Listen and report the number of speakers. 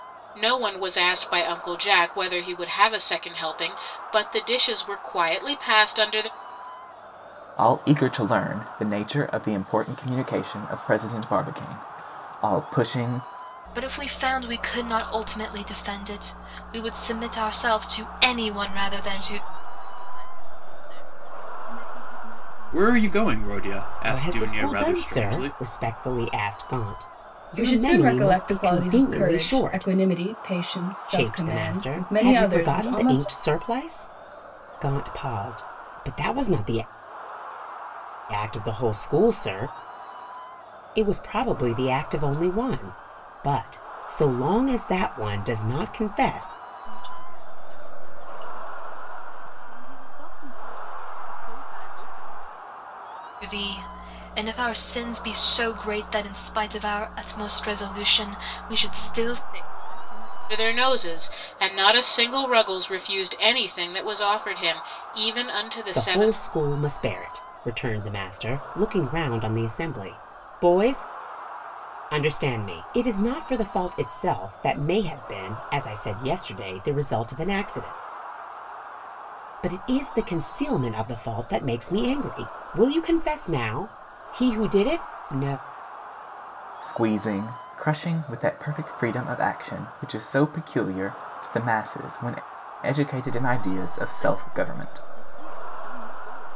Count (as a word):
seven